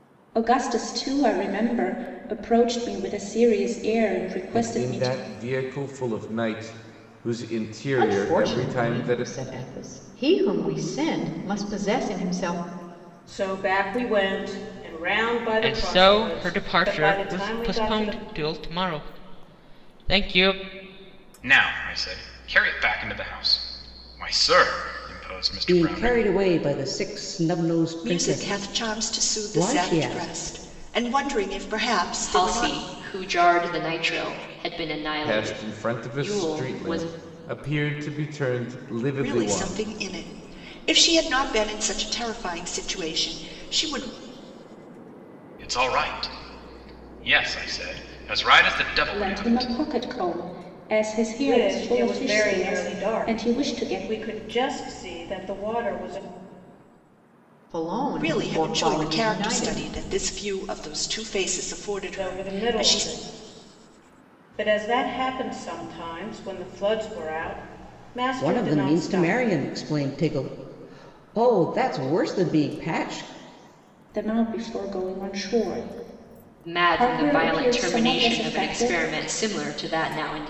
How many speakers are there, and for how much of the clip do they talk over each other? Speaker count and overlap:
nine, about 26%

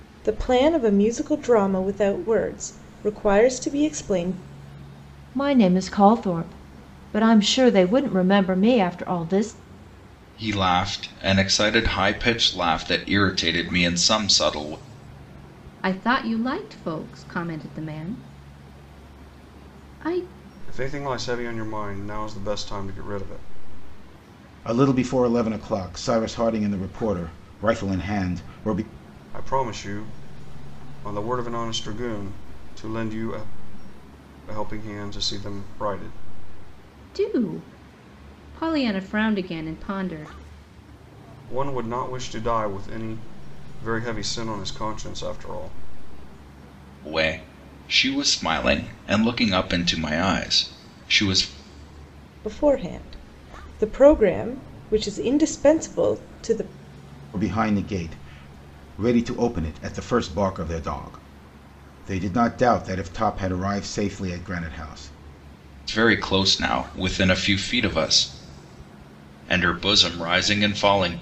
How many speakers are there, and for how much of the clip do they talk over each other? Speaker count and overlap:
six, no overlap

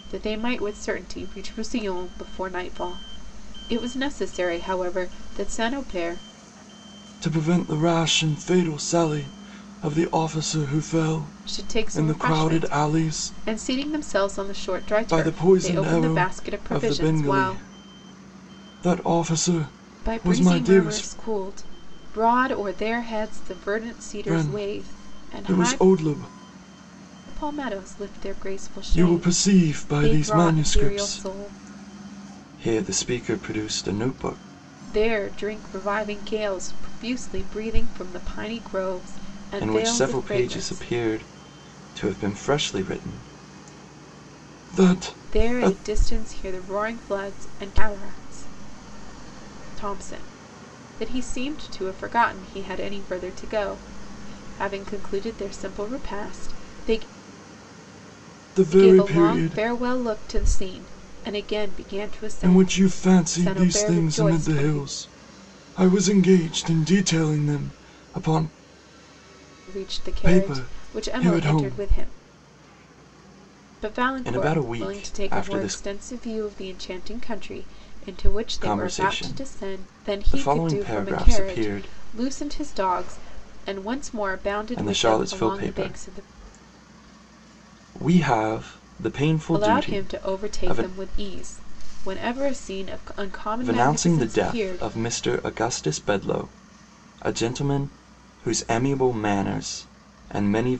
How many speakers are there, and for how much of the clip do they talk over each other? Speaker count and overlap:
two, about 27%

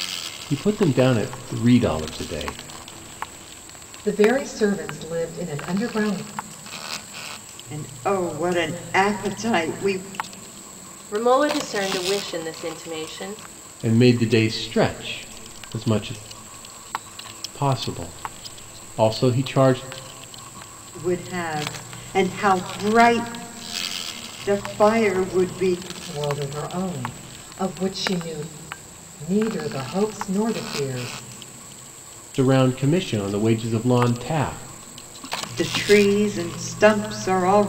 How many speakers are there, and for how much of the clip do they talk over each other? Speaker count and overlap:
four, no overlap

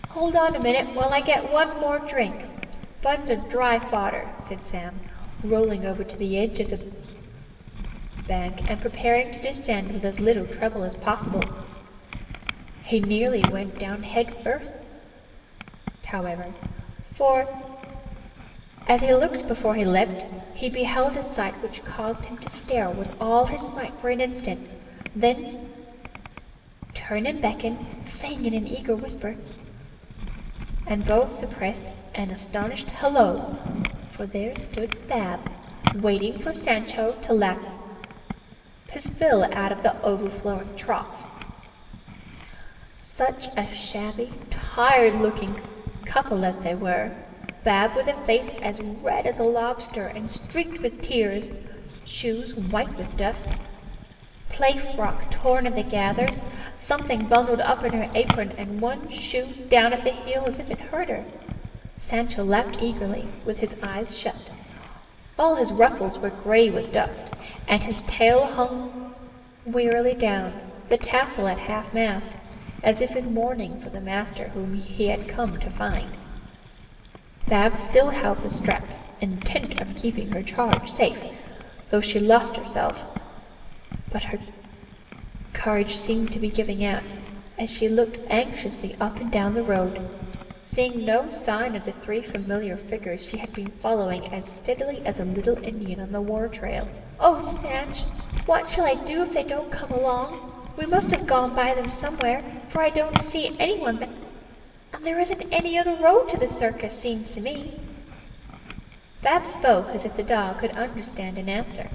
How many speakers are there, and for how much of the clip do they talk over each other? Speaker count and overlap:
one, no overlap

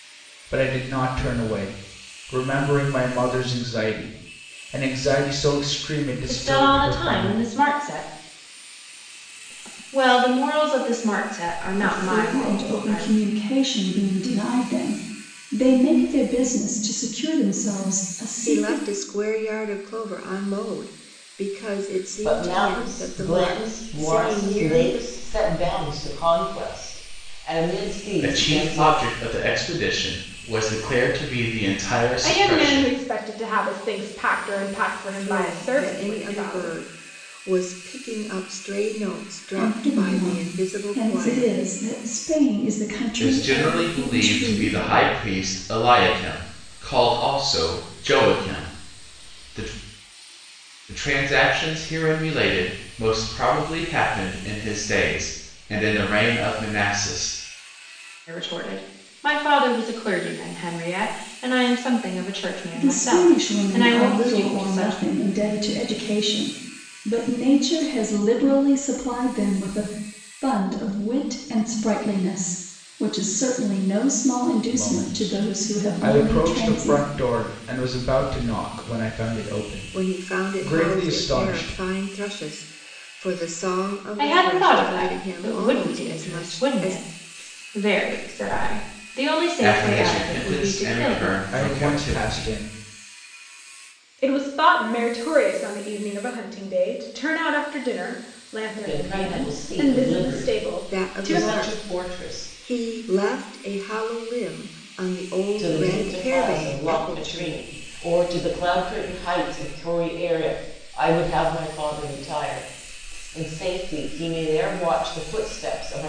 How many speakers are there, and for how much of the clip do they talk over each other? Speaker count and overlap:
seven, about 27%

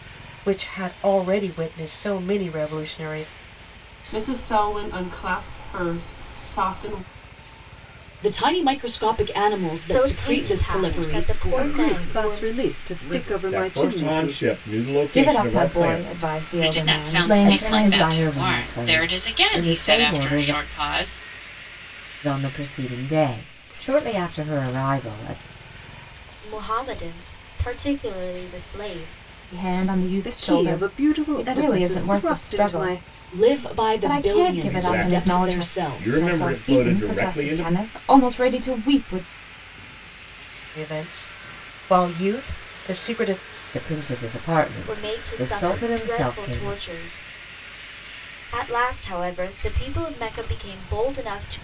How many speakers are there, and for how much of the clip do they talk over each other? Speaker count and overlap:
ten, about 37%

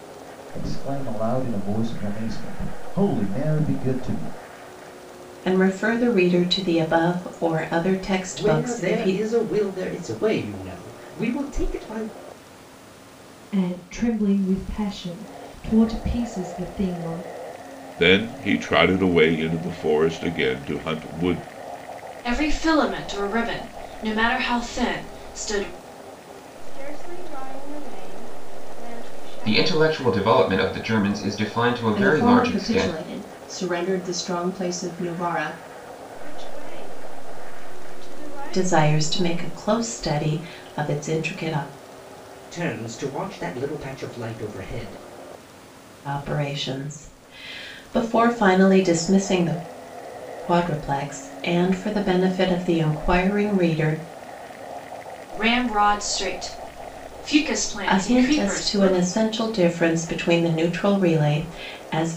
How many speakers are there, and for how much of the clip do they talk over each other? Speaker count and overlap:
nine, about 8%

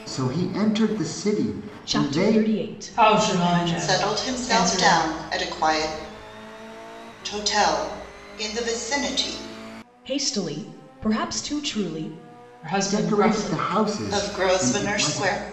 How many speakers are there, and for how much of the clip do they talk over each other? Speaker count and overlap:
four, about 31%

